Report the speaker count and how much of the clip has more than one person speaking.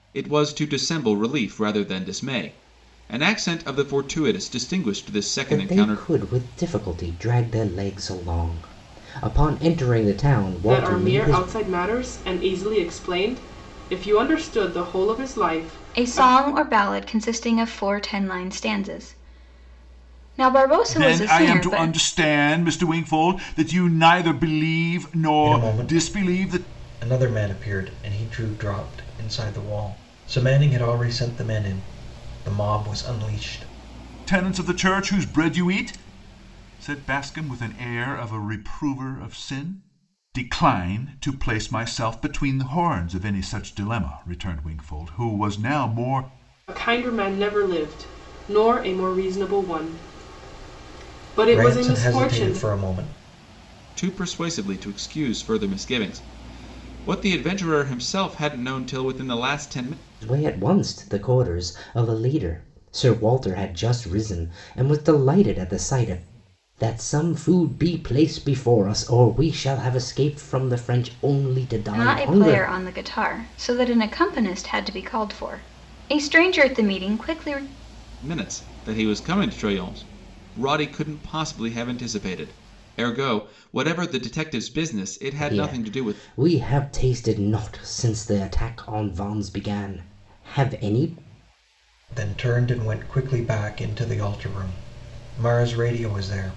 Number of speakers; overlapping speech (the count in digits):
6, about 7%